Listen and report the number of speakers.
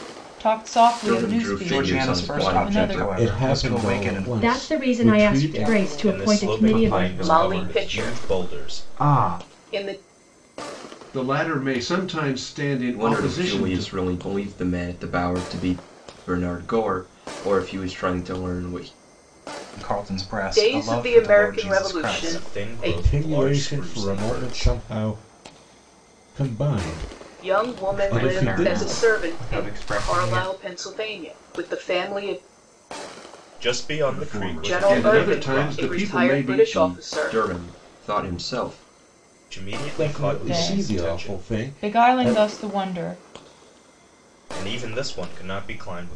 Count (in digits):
10